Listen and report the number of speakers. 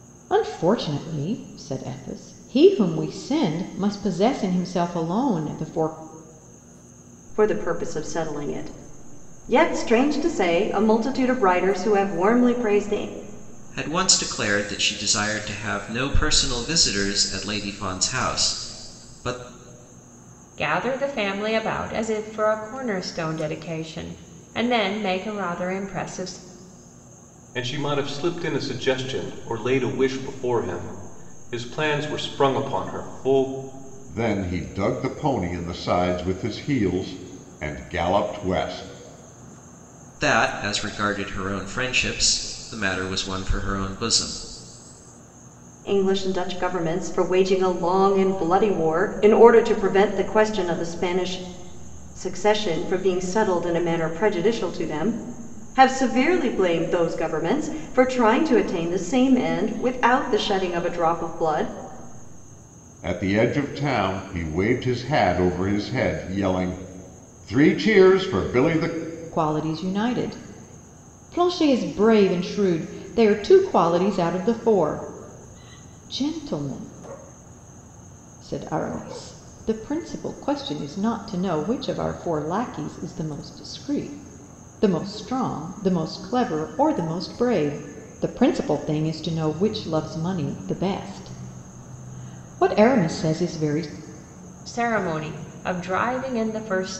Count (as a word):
six